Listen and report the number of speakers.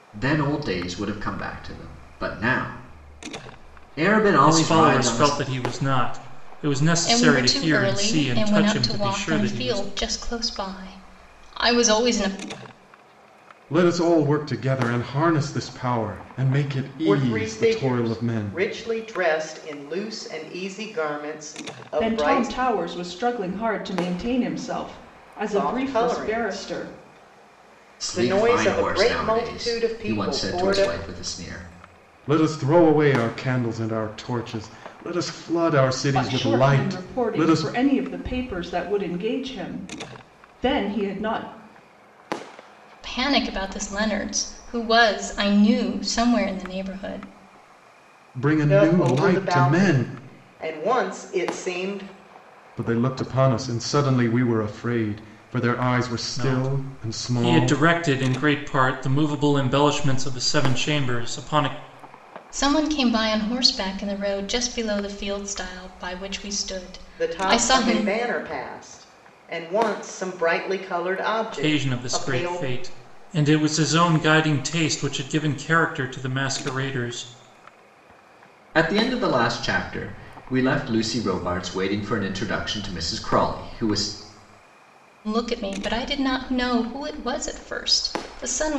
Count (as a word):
six